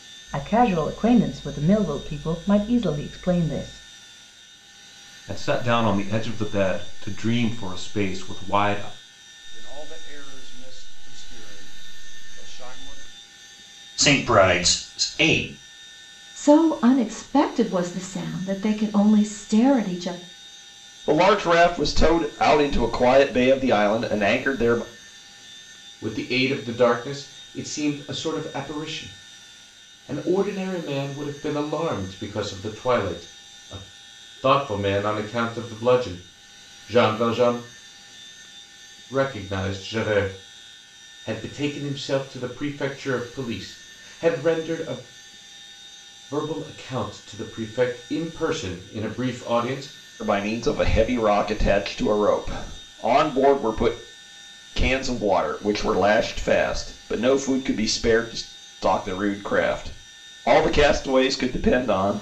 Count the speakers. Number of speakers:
7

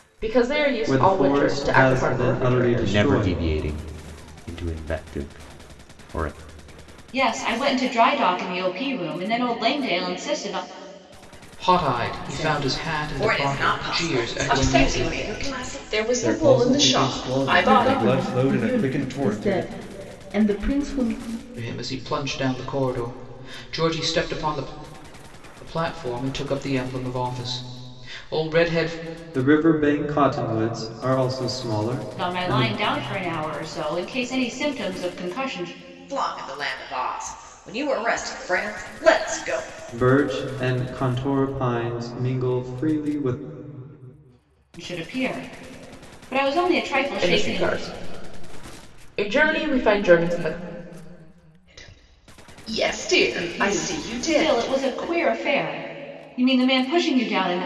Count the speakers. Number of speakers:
9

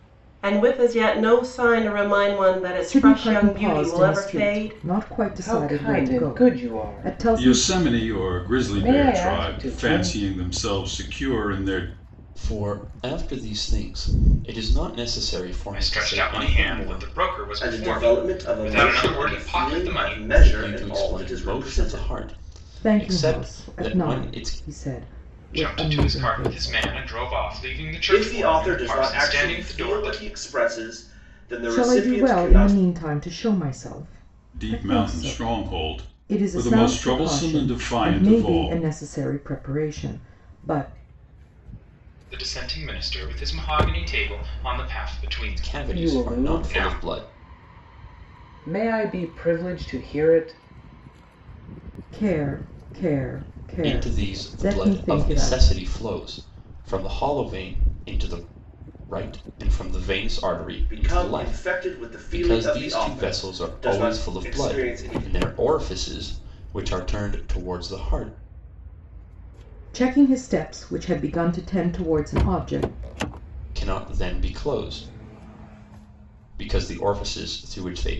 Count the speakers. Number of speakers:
7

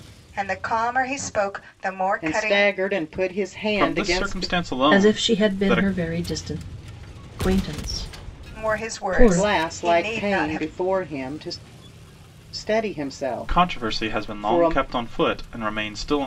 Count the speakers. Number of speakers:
4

